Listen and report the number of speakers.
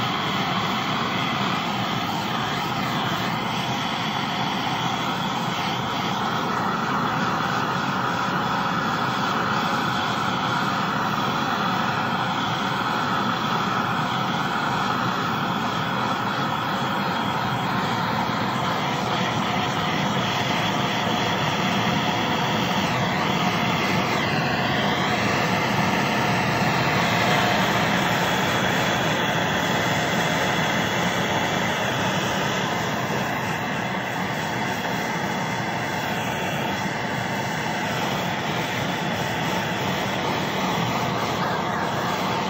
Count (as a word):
zero